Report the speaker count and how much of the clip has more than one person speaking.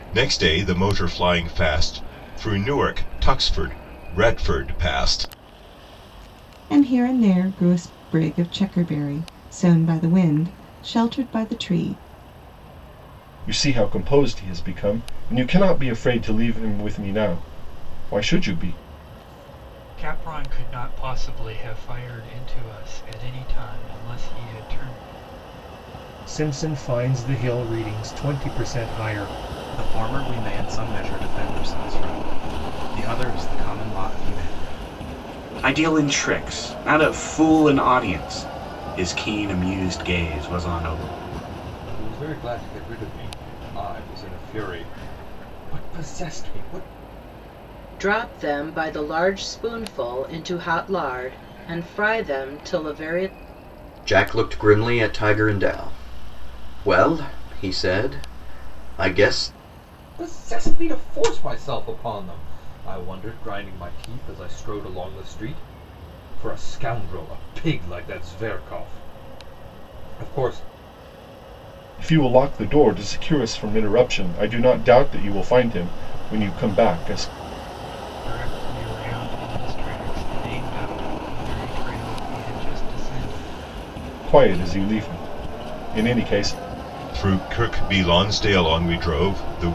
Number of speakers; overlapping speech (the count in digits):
10, no overlap